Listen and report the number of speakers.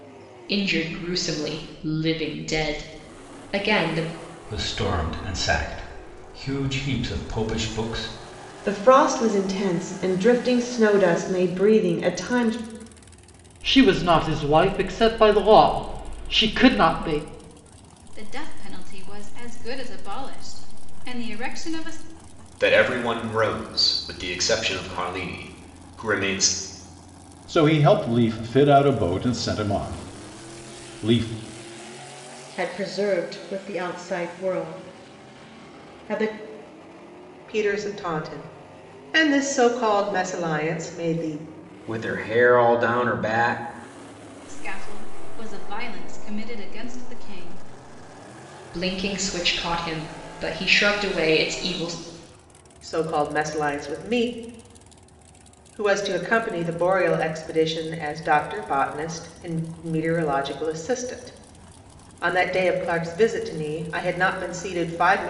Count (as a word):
ten